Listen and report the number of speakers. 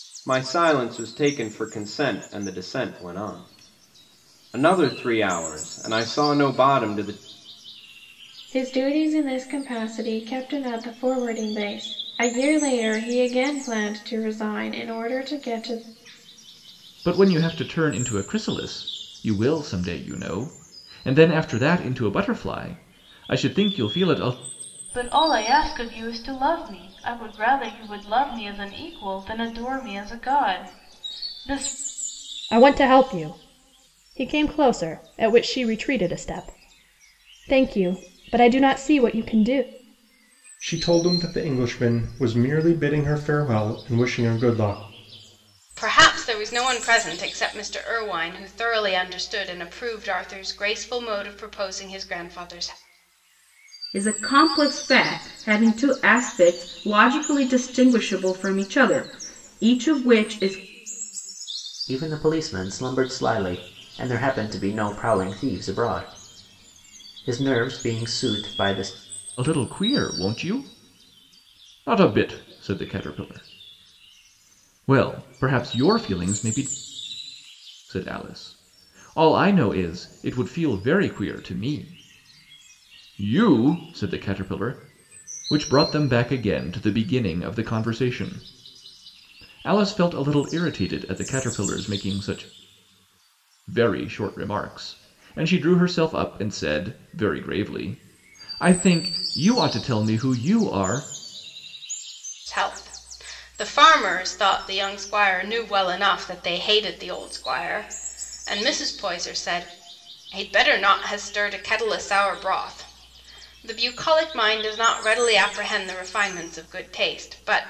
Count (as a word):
nine